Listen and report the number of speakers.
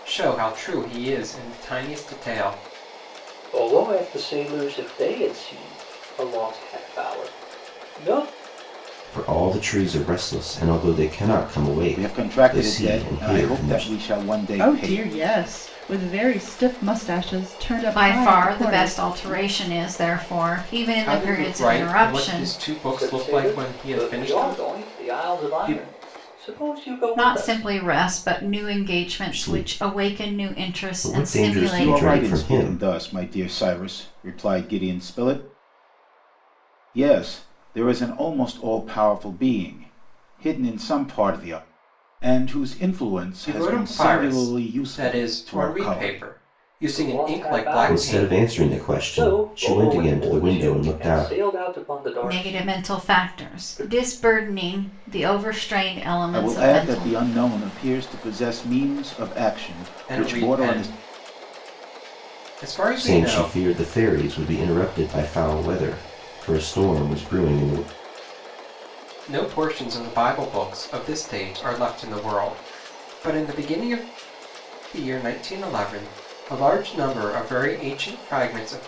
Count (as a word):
six